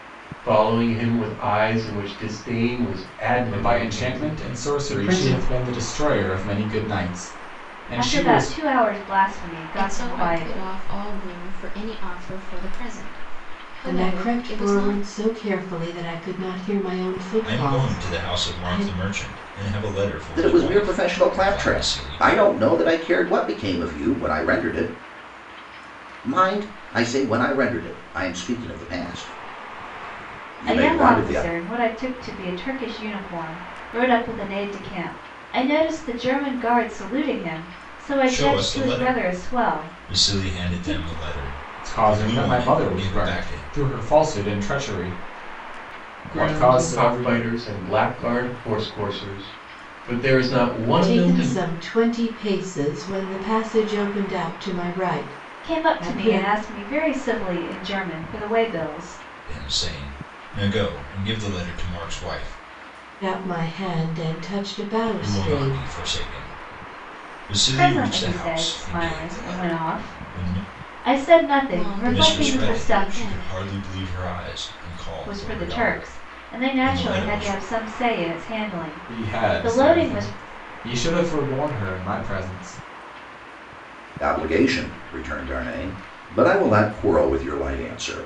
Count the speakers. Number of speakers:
7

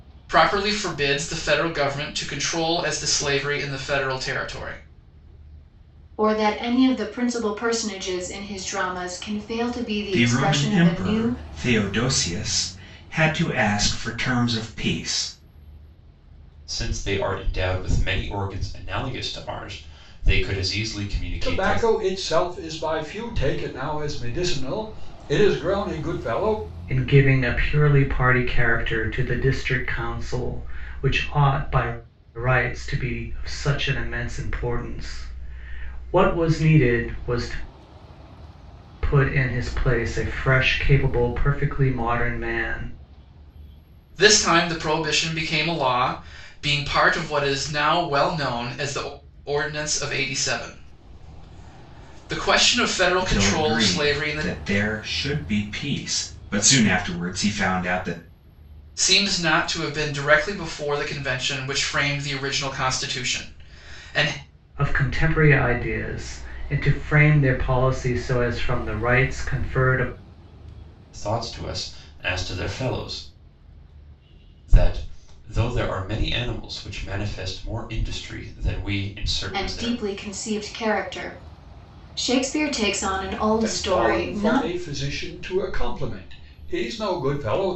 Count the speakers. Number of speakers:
6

